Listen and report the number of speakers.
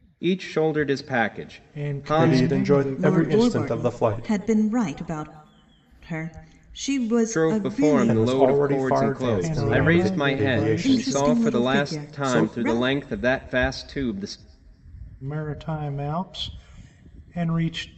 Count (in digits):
4